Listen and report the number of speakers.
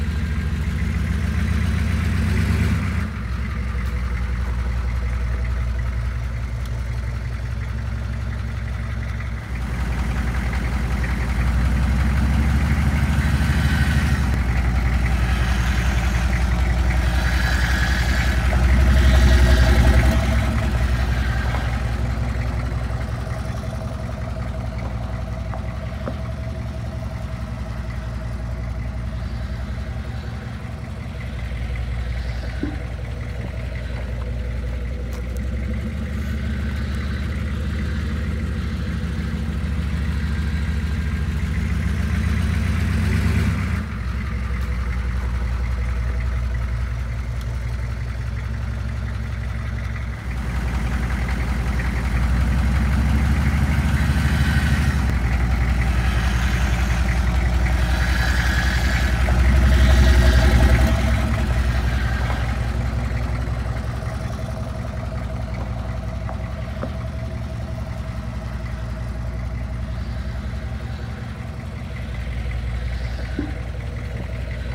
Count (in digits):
0